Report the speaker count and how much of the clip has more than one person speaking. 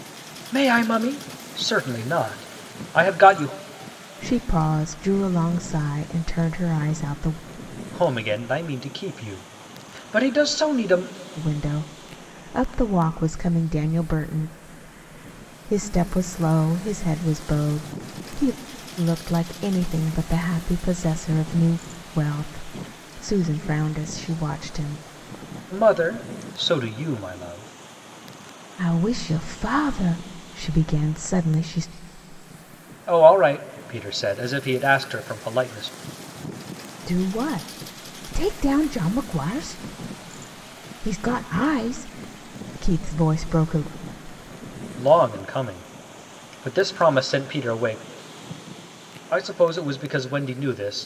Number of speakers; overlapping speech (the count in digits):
2, no overlap